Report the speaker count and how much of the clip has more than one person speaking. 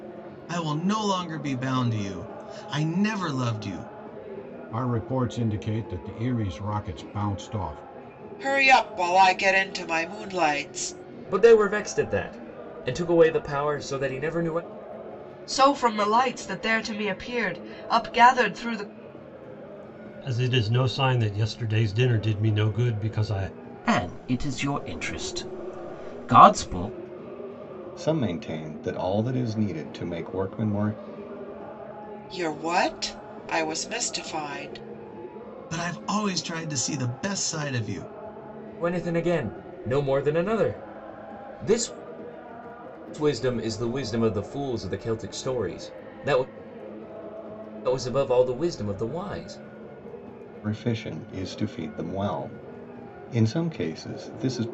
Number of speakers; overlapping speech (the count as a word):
eight, no overlap